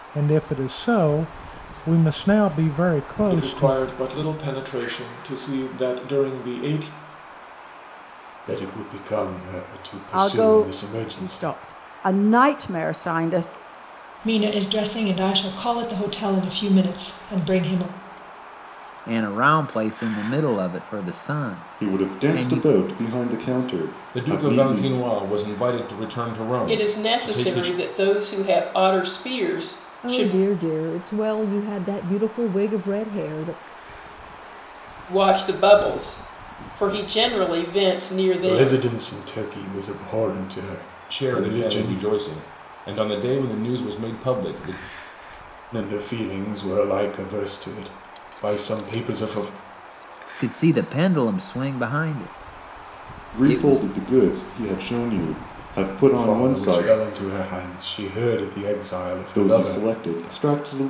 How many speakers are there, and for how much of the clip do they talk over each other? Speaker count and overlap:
10, about 14%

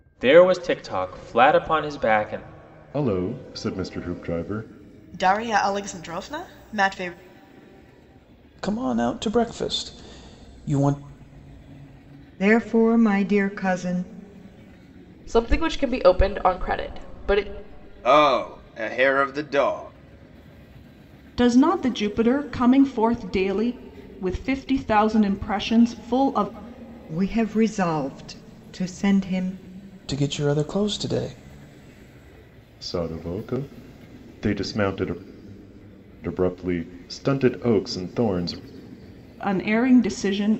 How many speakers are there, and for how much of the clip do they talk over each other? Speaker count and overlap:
8, no overlap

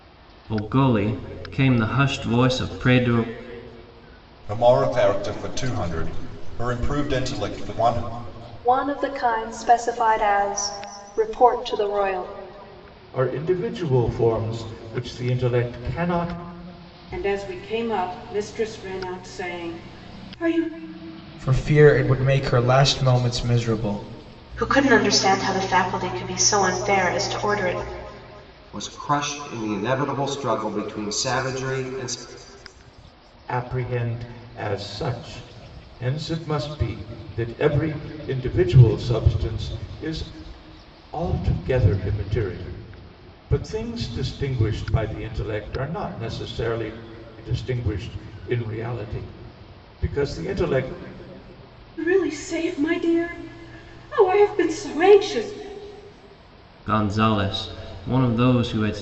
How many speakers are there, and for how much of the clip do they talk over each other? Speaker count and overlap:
8, no overlap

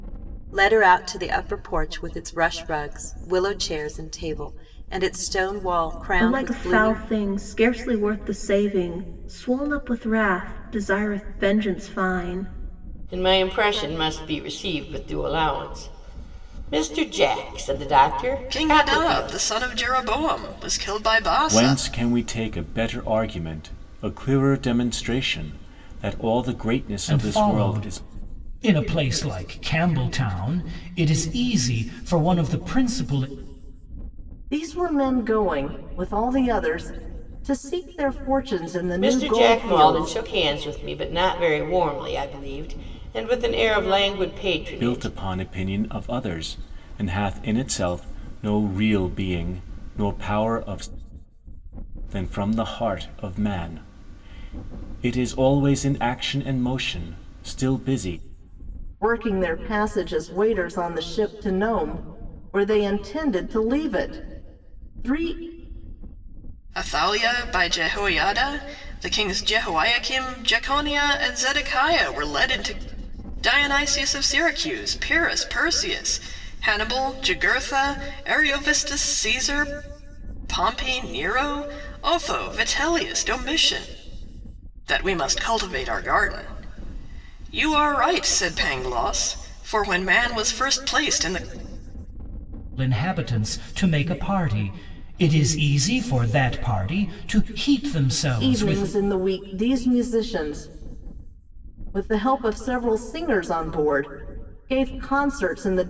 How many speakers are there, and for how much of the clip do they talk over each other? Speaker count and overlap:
7, about 5%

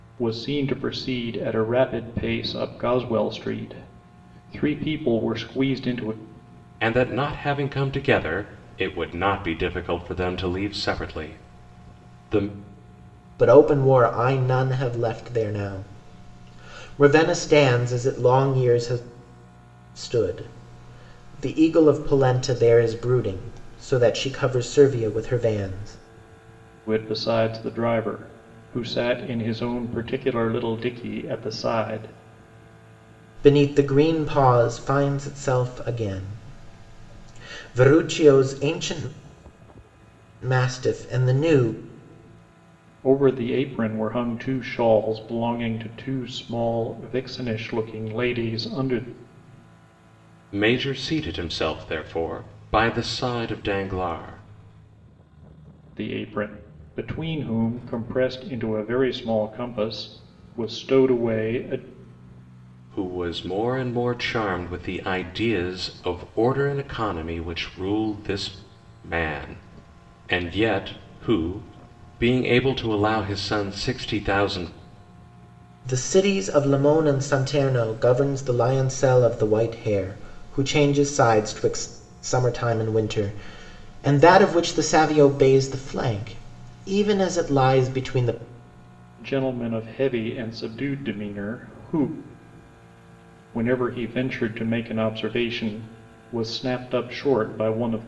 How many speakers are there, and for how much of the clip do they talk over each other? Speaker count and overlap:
3, no overlap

